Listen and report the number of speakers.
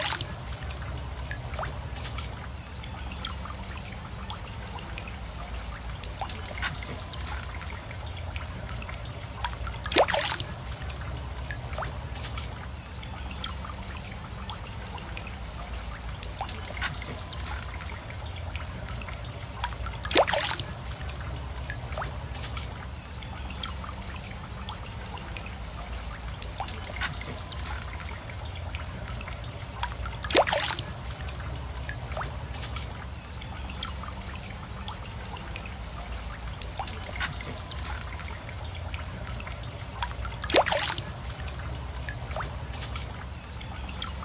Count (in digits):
0